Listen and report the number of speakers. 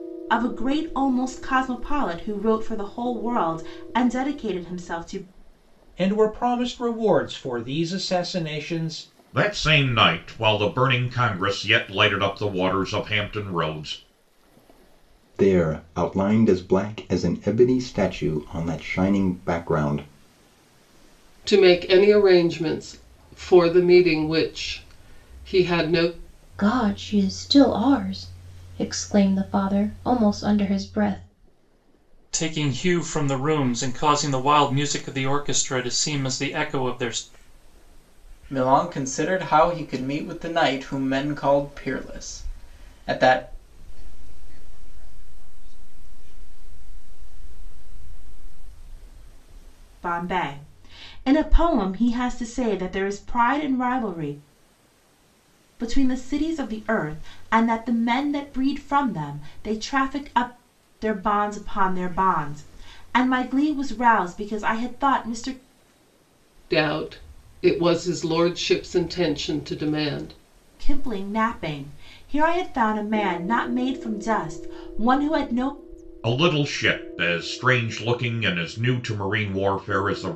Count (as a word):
nine